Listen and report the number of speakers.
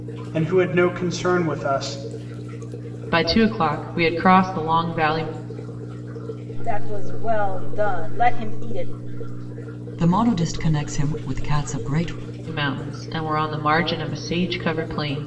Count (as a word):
four